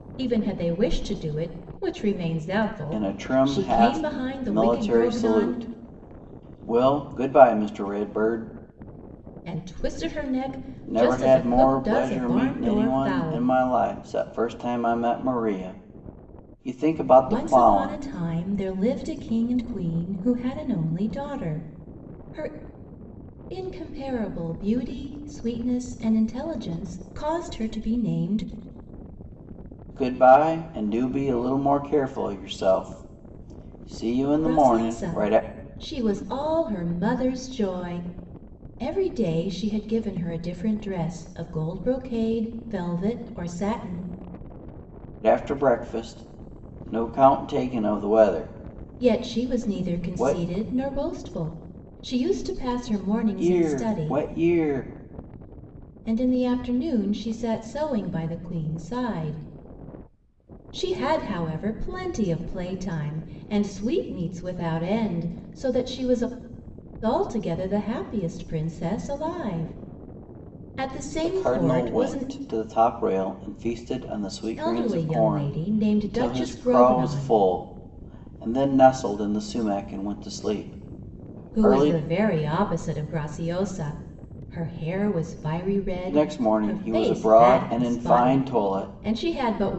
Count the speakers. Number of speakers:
2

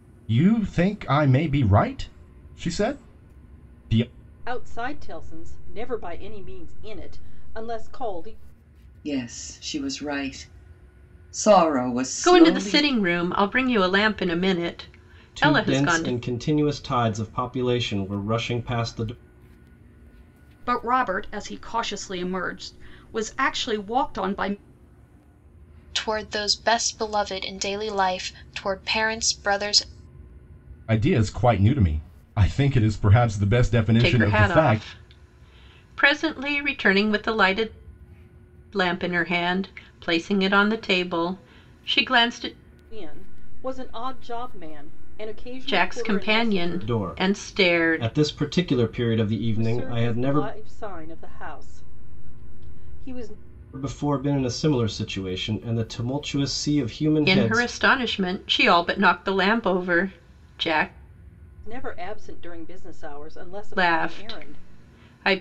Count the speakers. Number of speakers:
7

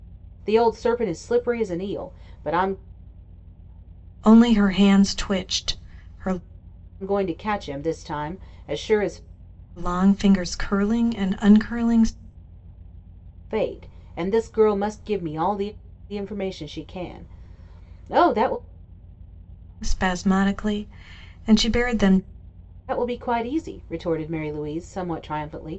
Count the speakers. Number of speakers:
2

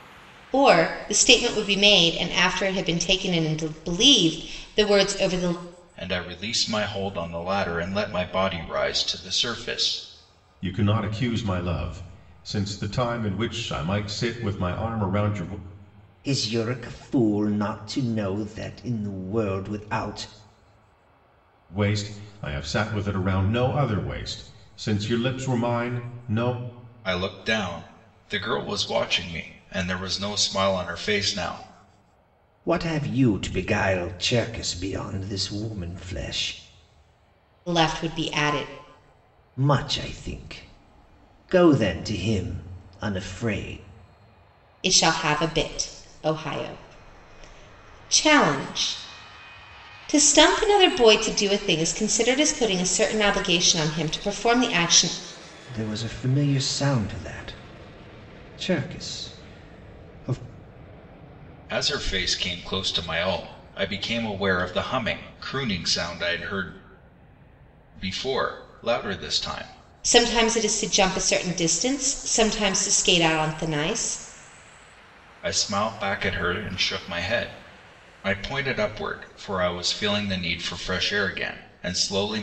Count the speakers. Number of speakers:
4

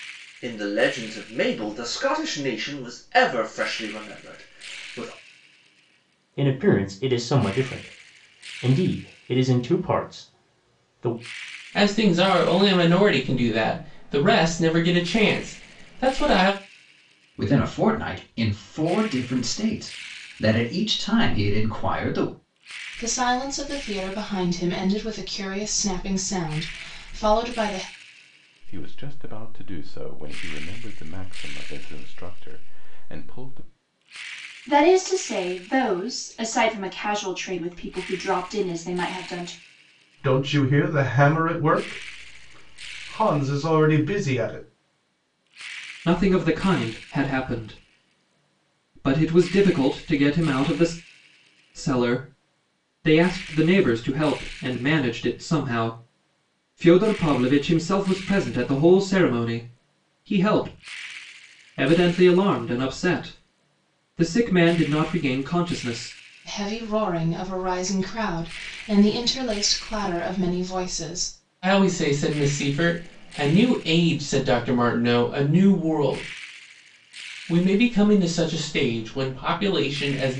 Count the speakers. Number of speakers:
9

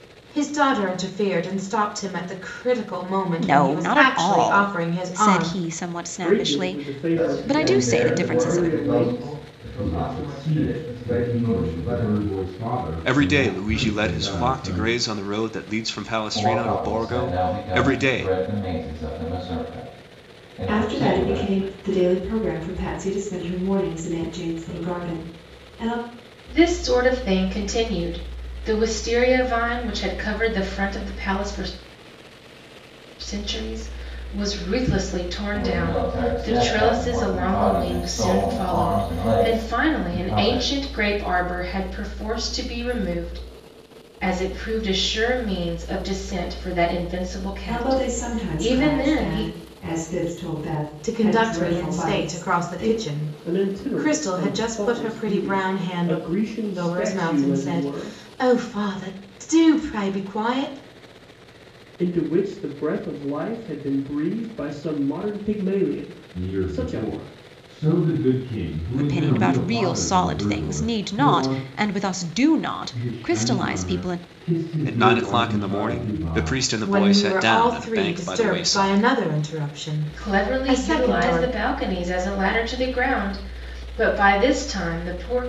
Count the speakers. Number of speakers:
9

